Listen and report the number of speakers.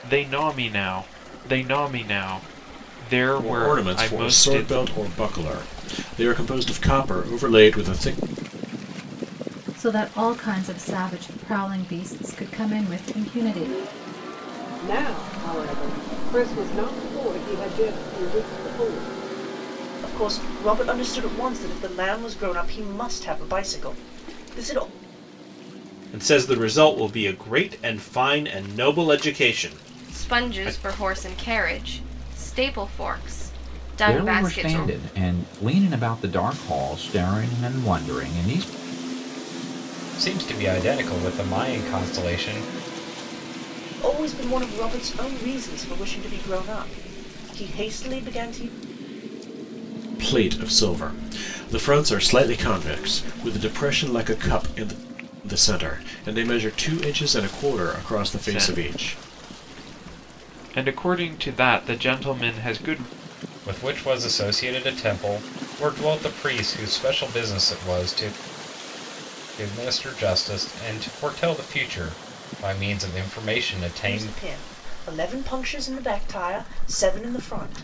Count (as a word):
nine